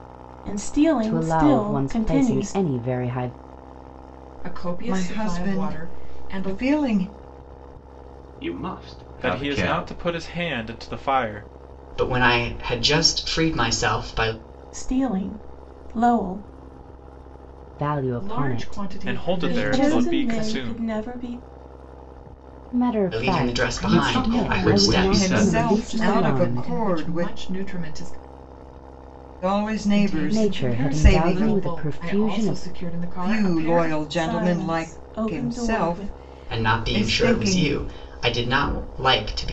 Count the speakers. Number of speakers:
7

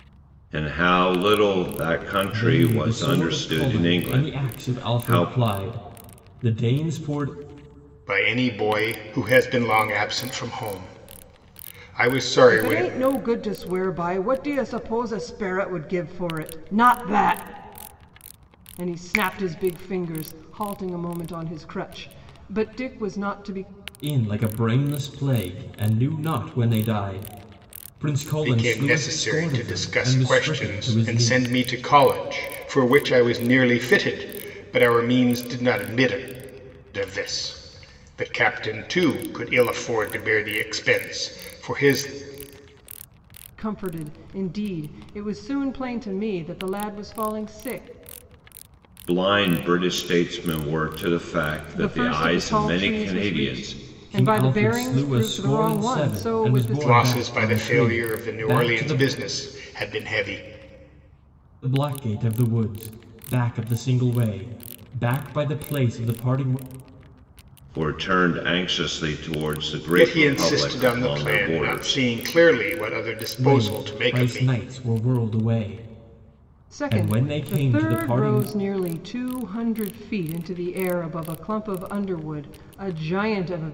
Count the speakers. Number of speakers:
4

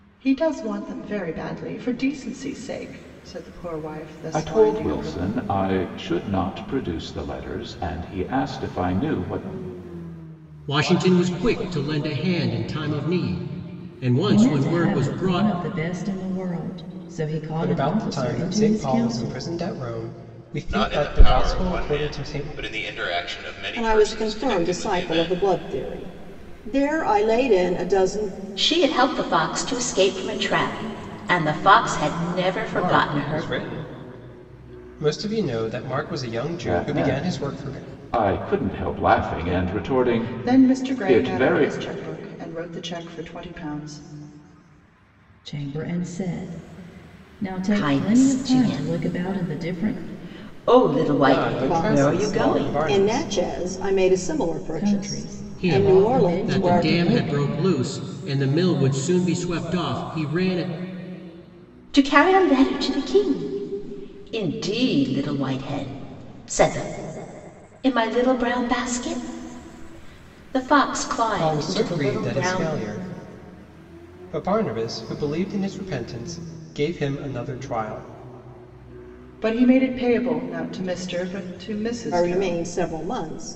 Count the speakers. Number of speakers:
8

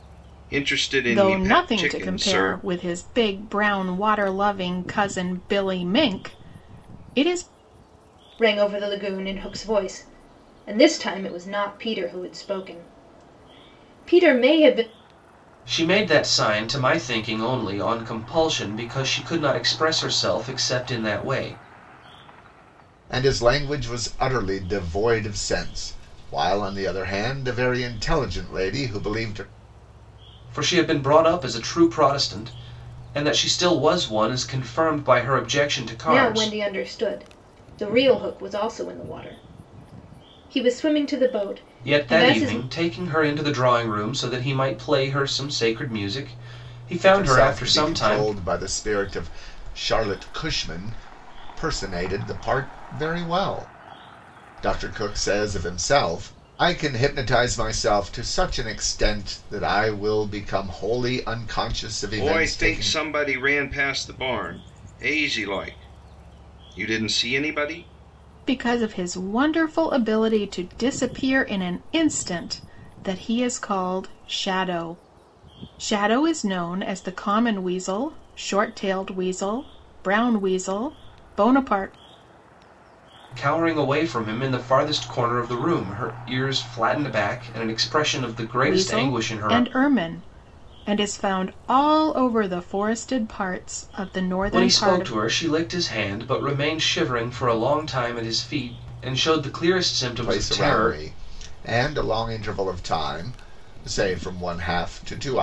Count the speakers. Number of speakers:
5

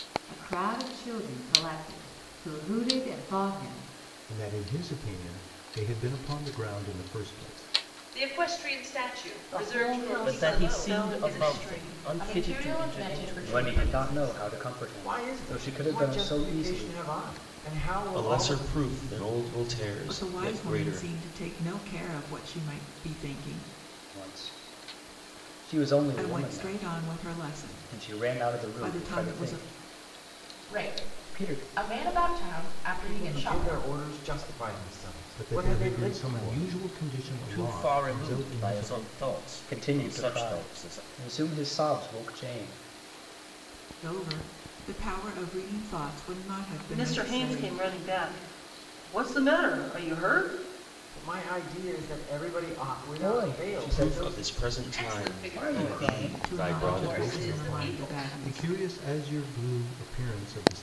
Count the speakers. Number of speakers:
10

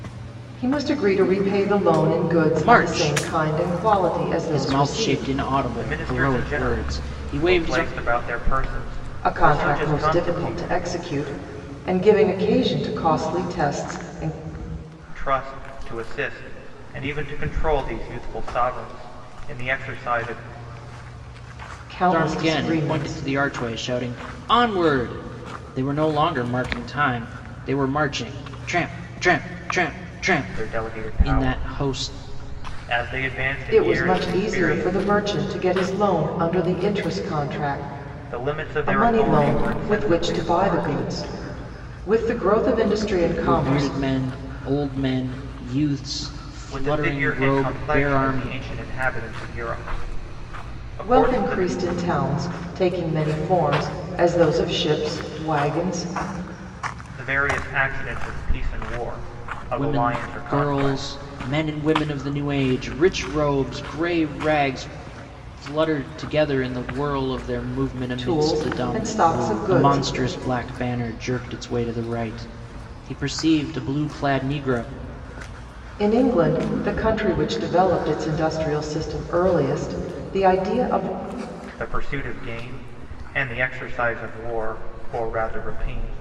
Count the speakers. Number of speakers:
3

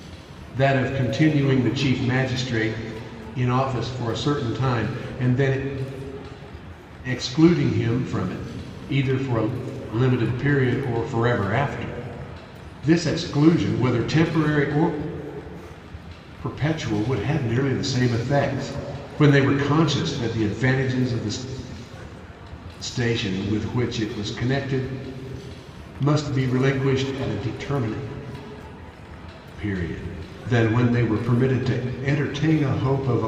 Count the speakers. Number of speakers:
1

